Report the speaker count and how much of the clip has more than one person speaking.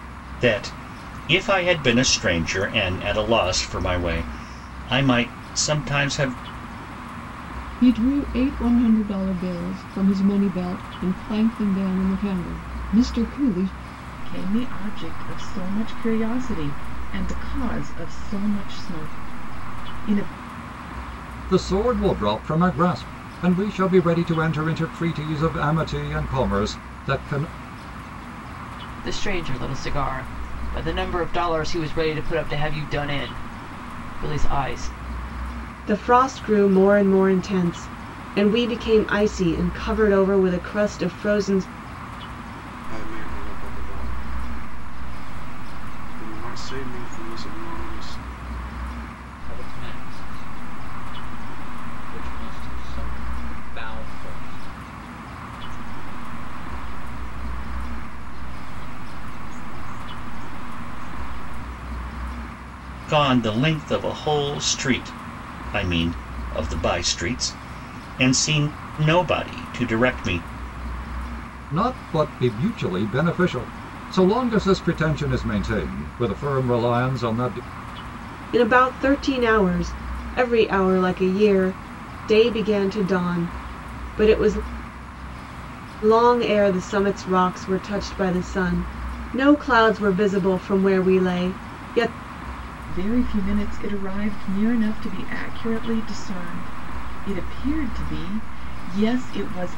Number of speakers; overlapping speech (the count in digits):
9, no overlap